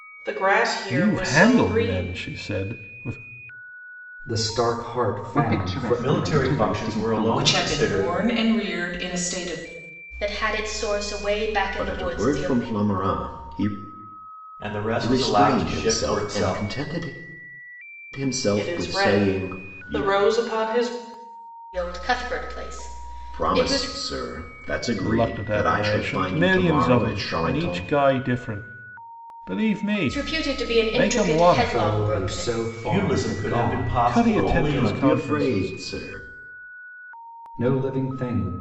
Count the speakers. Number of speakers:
eight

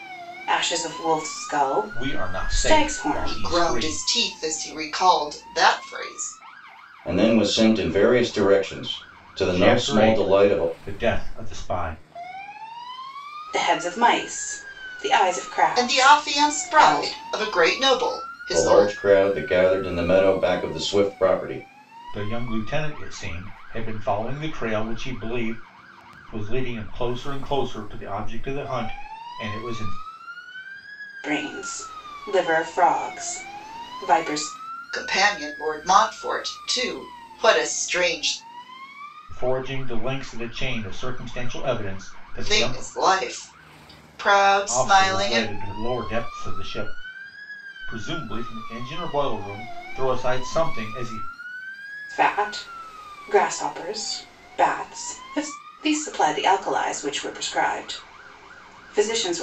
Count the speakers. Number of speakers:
four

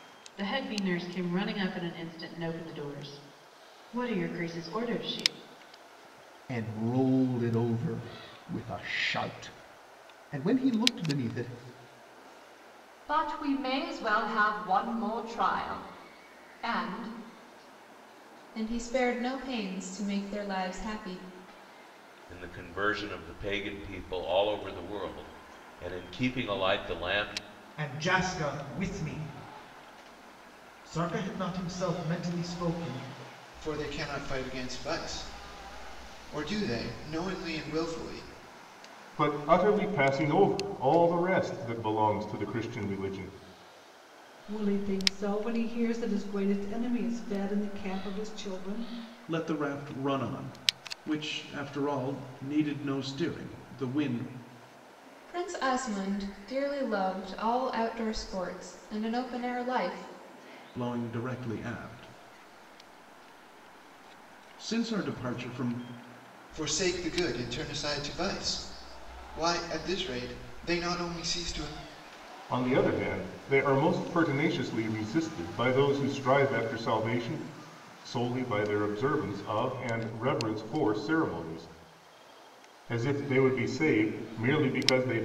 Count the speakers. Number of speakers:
ten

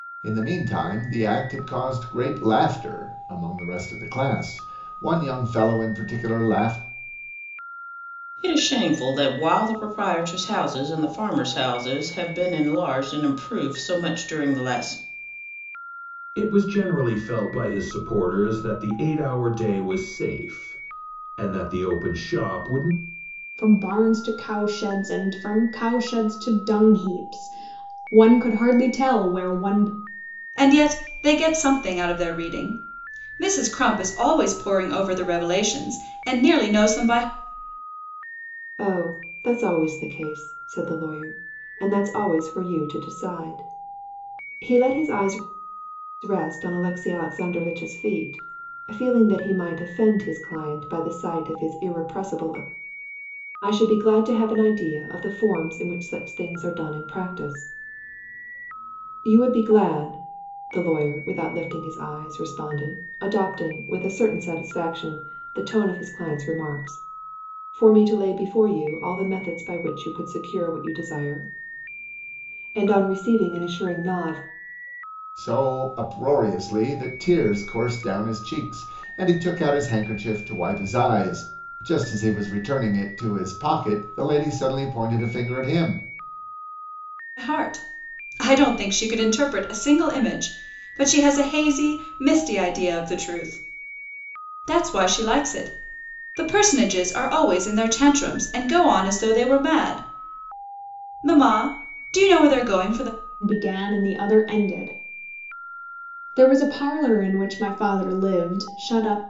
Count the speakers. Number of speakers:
six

